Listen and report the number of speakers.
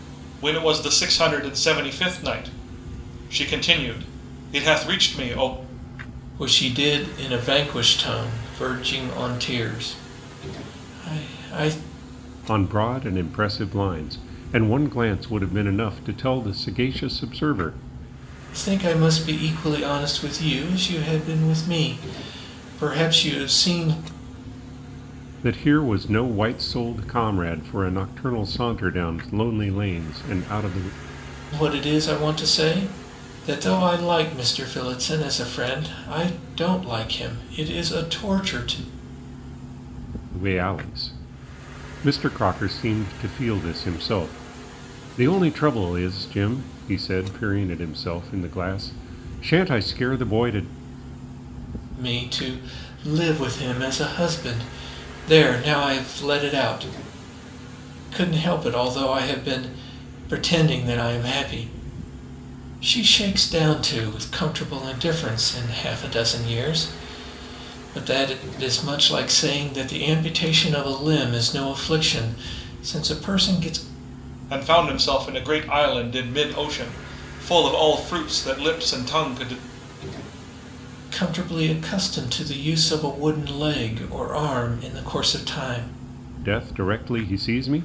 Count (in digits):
3